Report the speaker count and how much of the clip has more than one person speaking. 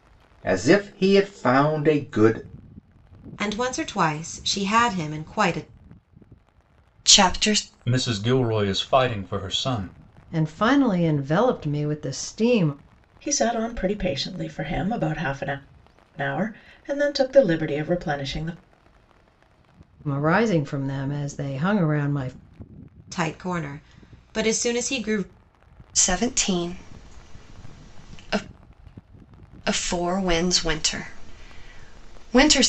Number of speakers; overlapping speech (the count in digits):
6, no overlap